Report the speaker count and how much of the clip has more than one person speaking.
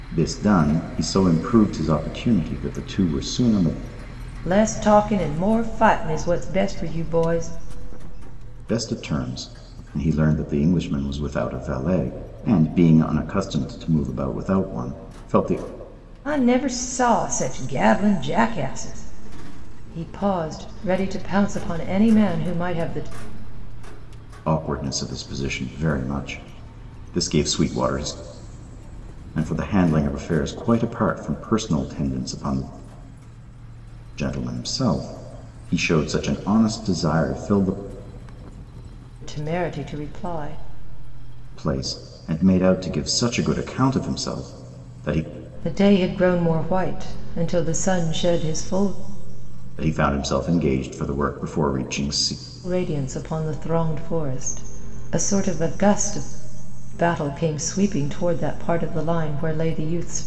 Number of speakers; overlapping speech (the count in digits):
2, no overlap